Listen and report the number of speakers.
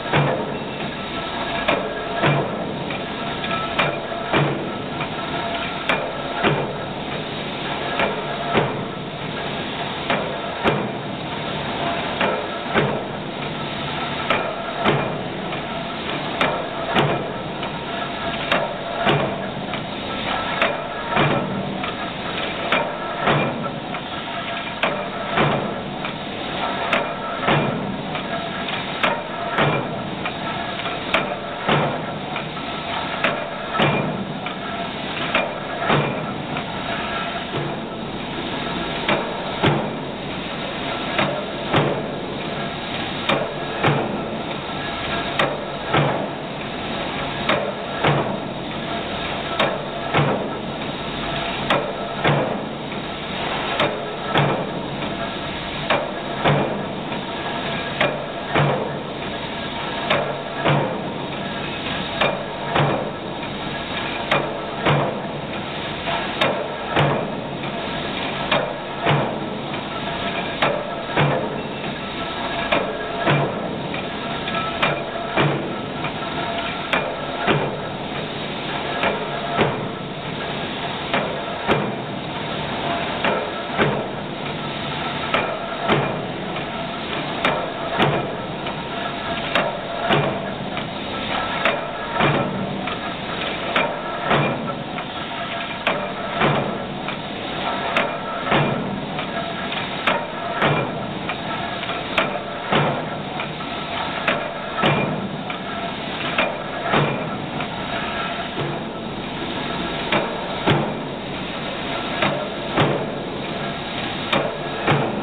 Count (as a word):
zero